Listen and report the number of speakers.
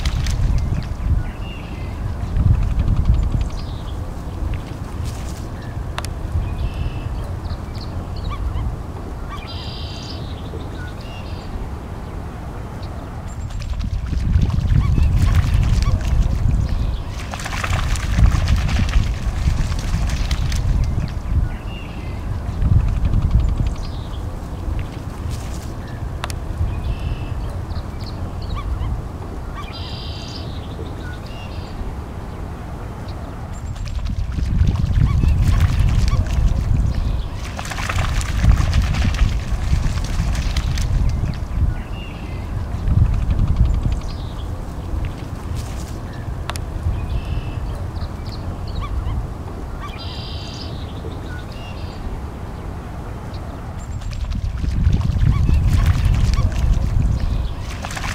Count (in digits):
0